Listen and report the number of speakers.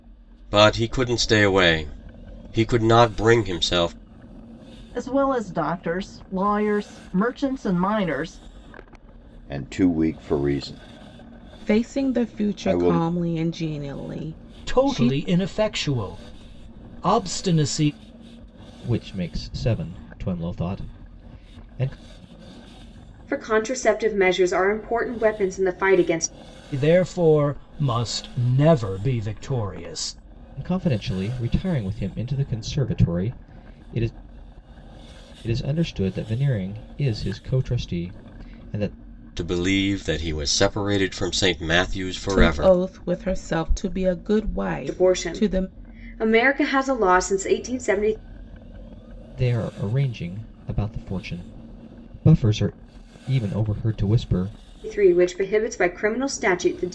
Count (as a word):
seven